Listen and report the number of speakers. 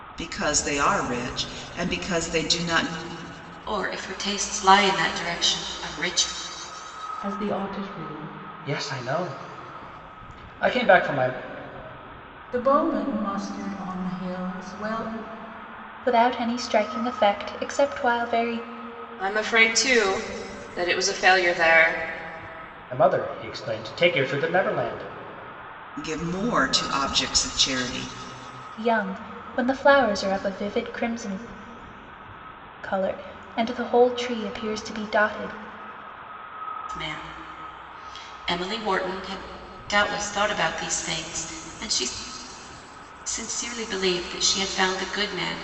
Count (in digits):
7